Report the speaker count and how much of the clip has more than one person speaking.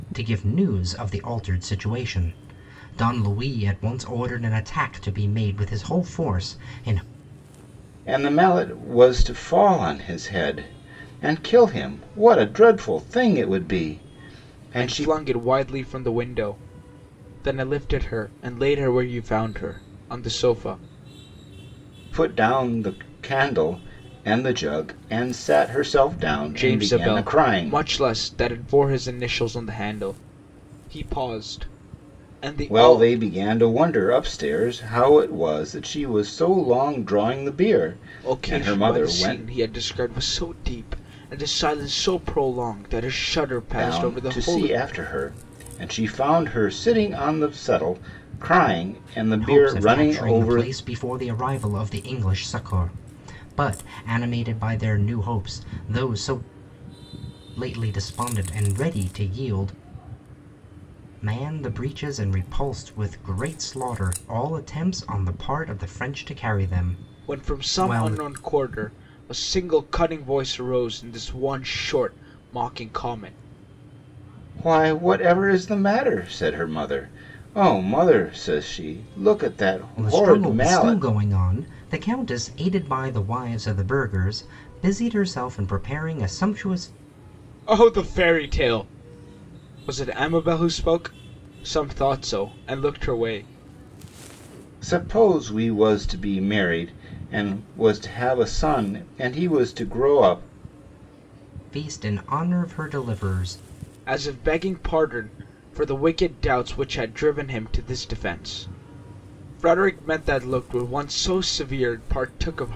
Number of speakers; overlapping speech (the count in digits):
3, about 7%